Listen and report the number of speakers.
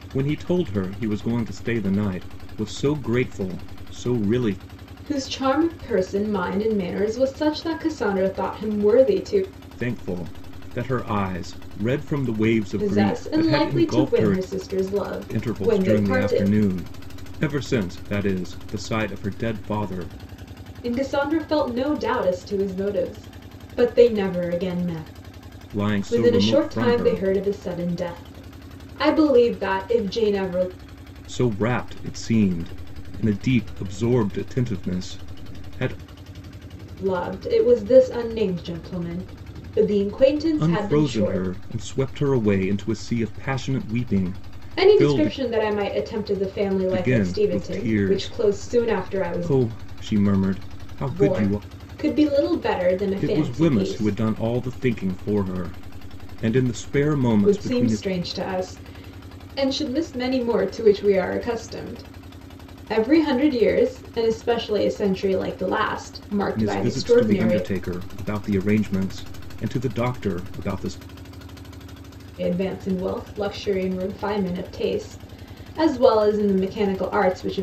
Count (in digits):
2